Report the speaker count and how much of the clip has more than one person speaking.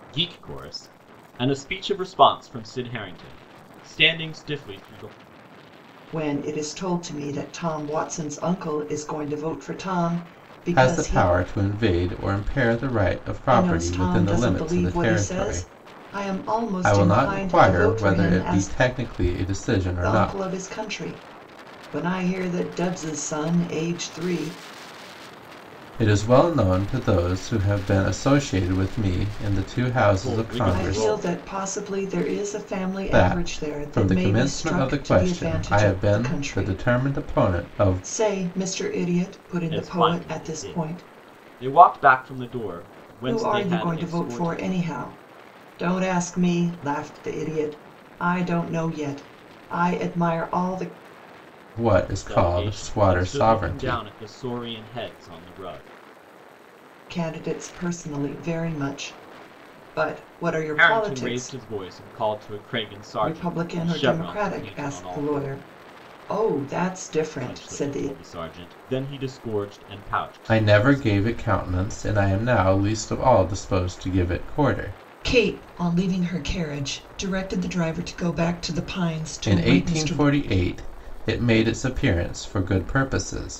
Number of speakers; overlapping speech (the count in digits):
3, about 26%